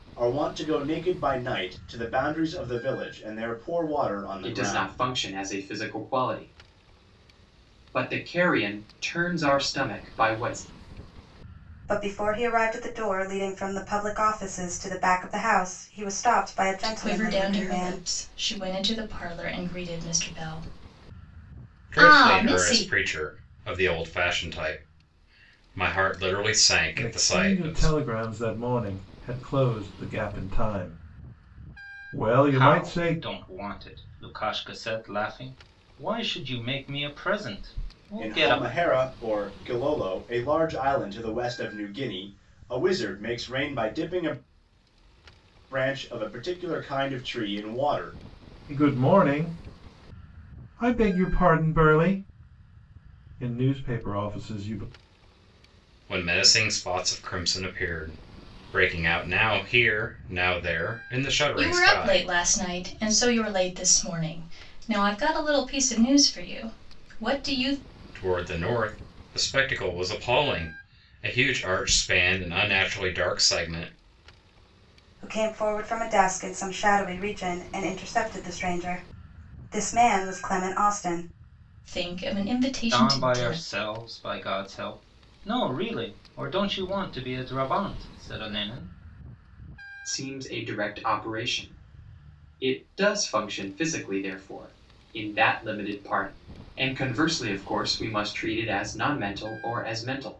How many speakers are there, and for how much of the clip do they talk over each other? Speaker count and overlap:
7, about 7%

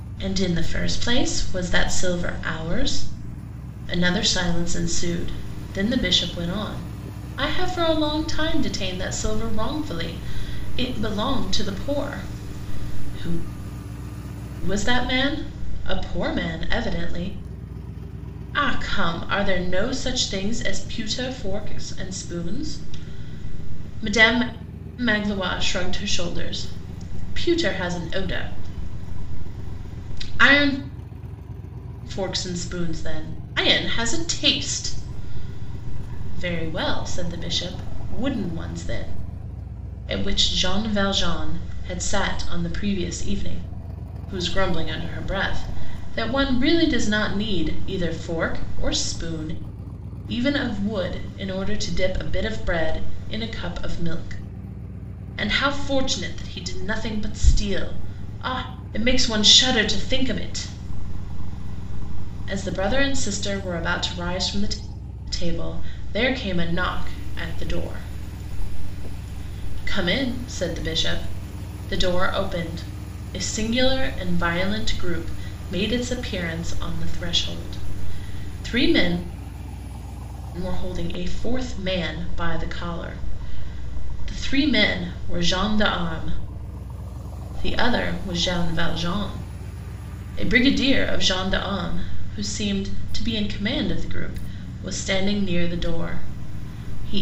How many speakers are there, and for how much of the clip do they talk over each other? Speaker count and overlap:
1, no overlap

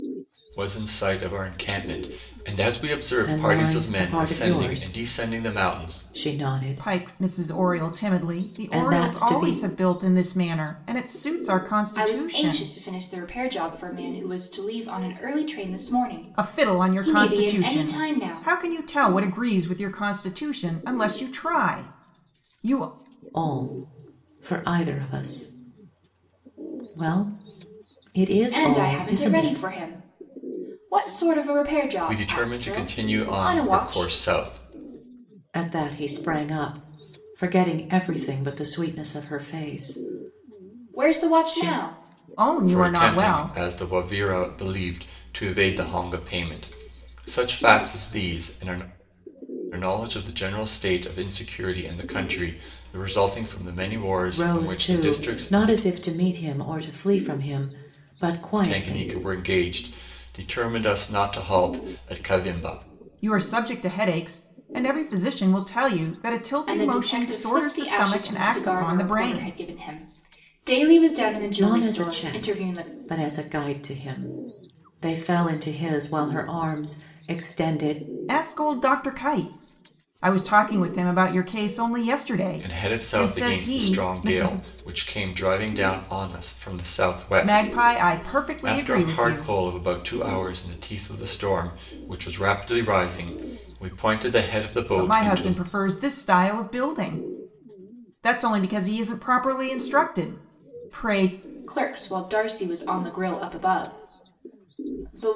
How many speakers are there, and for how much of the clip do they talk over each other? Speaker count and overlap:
4, about 23%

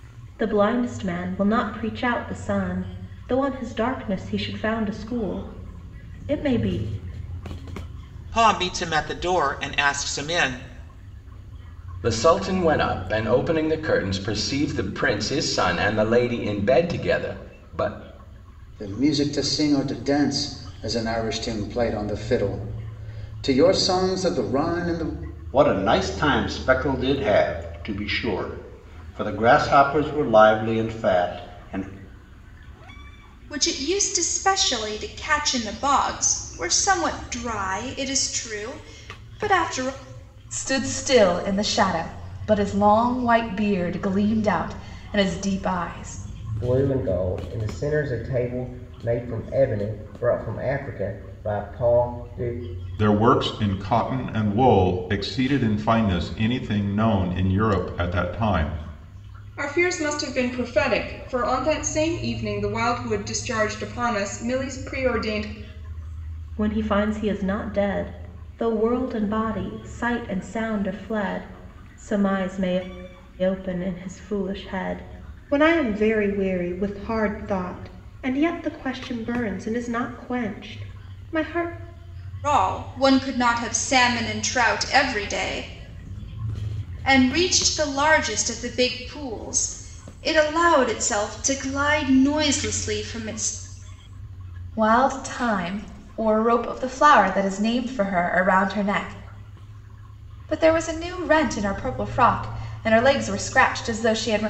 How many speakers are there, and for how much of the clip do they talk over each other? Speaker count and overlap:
10, no overlap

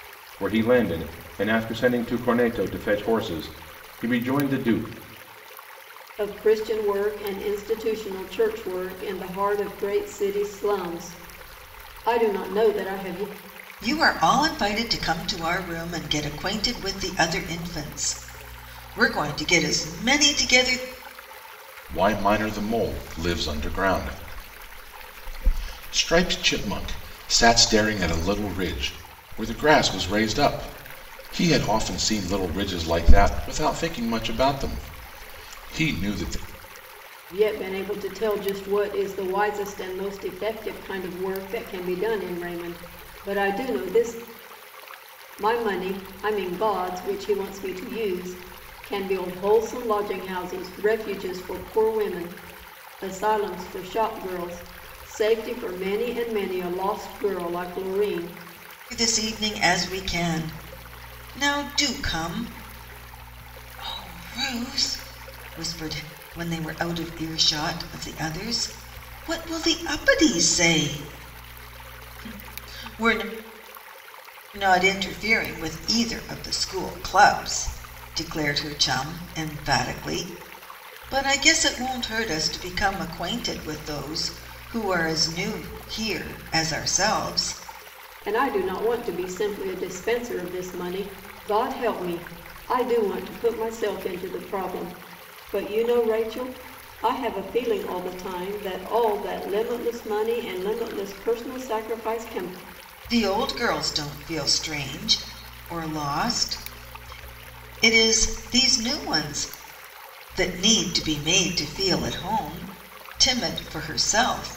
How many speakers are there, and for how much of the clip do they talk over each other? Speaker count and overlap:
3, no overlap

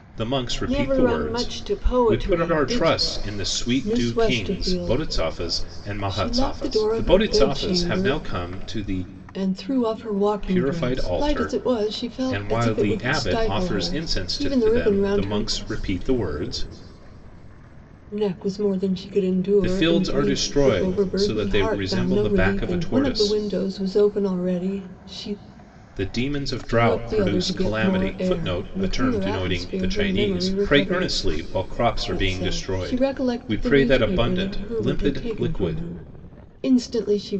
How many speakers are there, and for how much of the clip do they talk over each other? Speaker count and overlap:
2, about 58%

